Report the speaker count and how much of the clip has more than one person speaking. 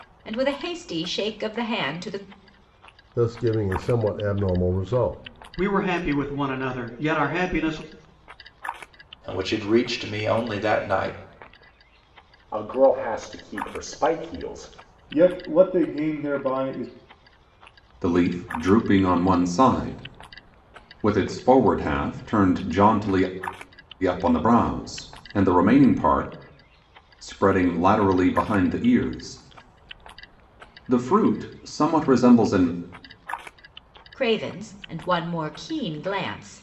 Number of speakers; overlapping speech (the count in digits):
7, no overlap